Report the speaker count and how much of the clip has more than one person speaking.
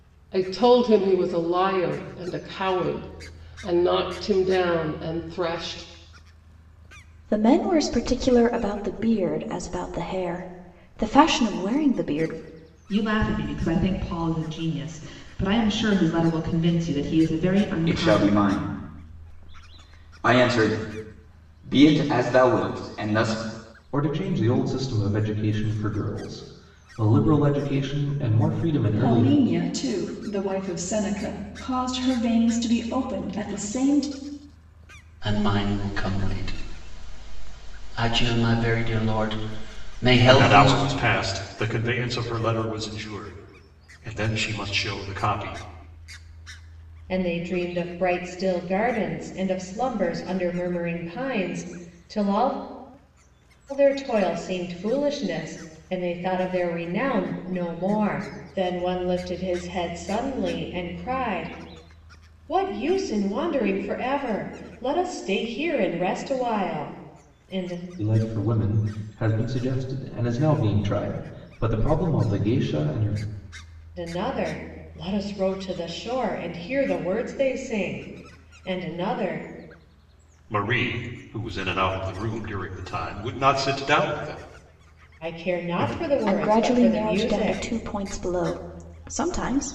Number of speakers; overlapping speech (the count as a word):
nine, about 4%